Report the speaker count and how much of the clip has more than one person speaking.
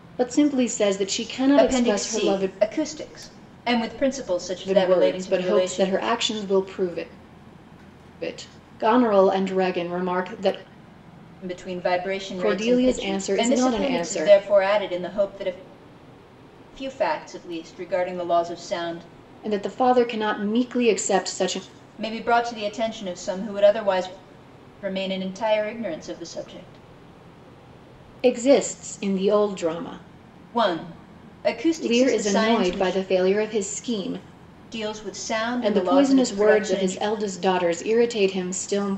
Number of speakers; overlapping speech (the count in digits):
2, about 18%